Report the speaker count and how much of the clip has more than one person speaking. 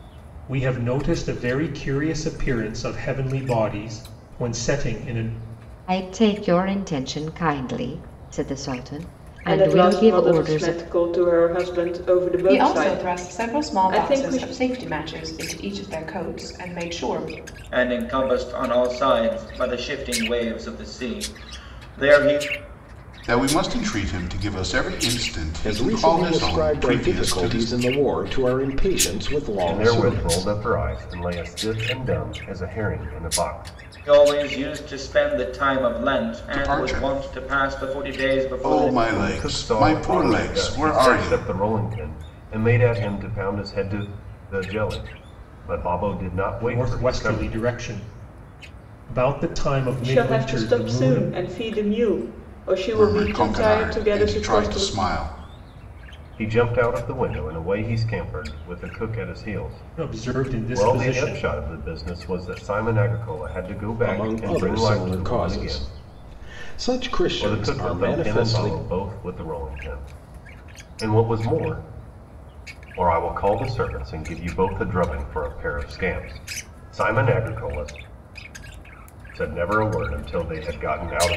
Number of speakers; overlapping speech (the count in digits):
8, about 25%